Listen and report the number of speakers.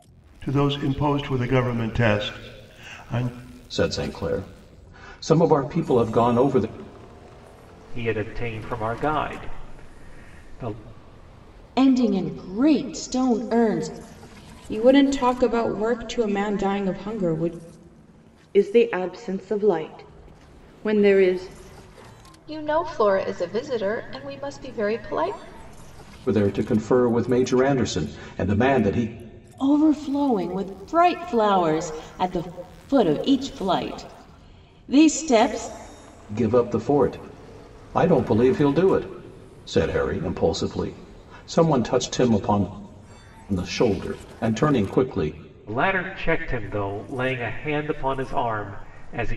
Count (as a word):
seven